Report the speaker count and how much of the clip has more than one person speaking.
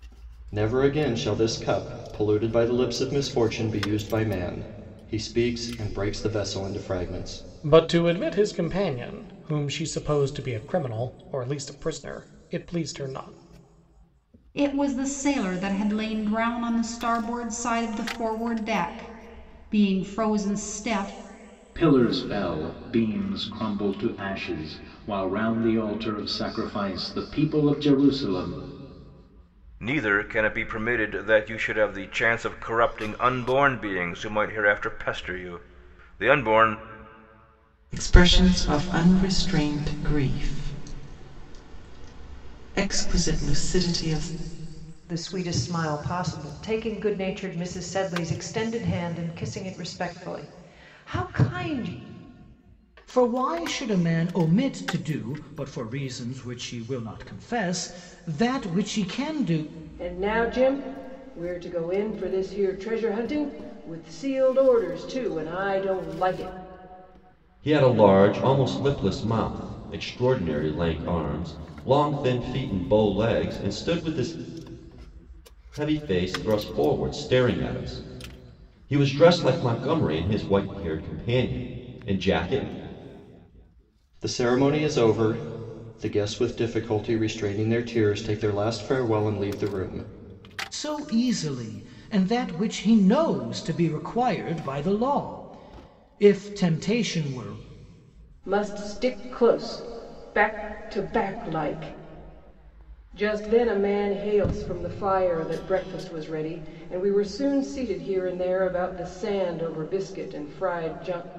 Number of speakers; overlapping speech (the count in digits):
10, no overlap